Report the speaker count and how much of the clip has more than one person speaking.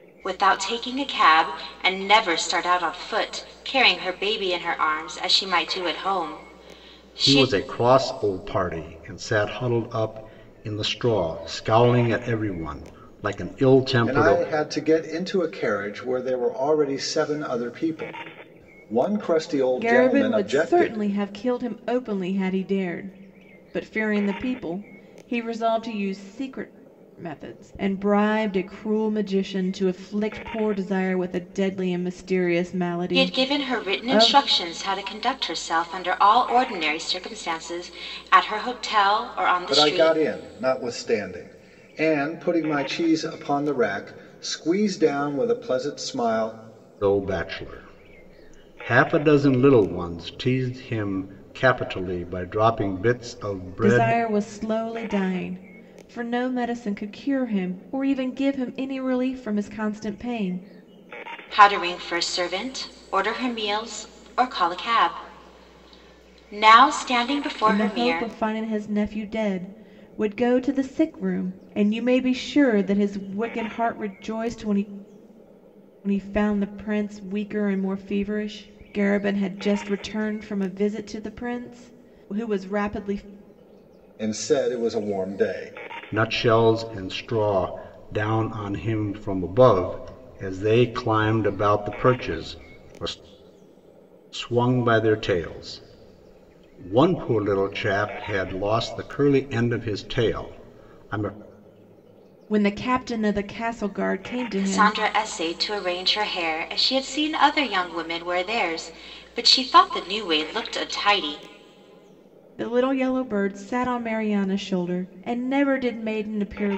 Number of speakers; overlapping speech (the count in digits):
4, about 5%